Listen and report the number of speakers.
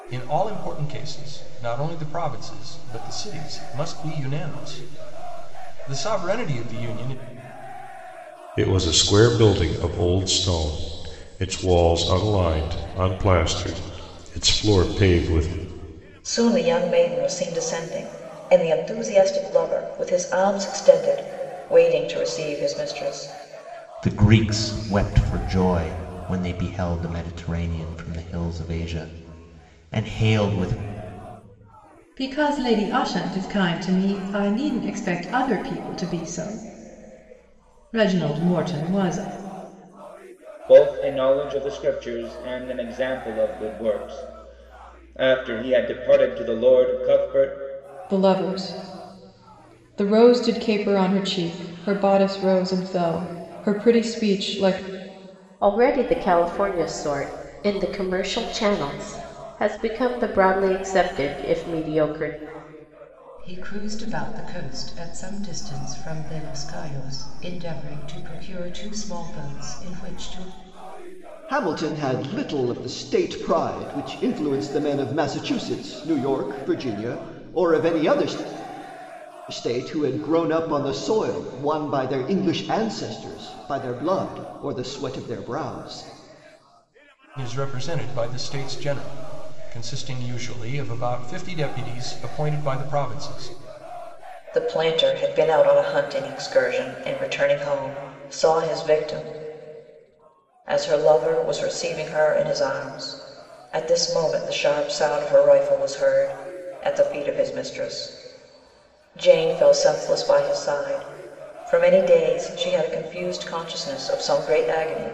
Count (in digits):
10